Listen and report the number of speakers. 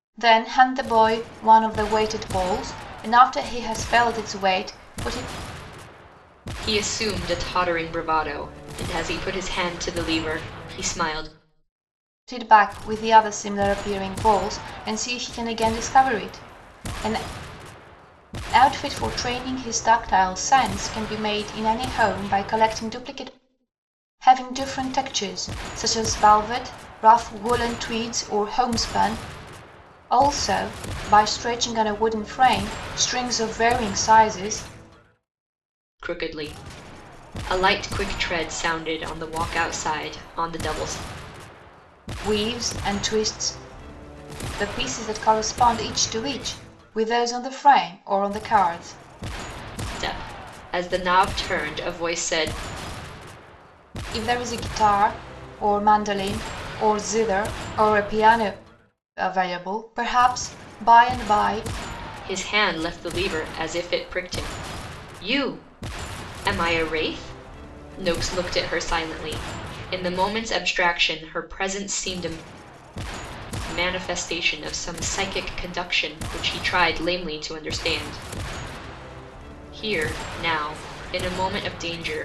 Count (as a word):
two